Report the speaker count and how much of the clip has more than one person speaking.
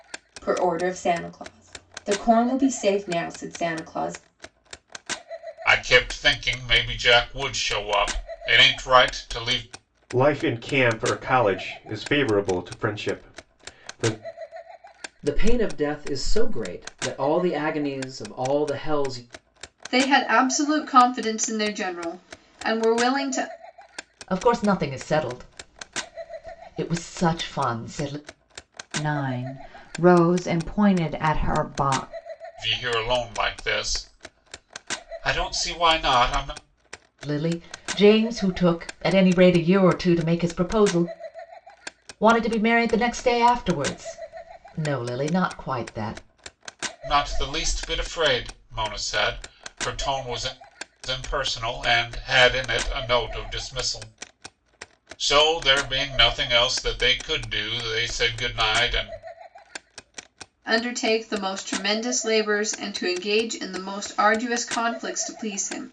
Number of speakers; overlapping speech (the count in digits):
7, no overlap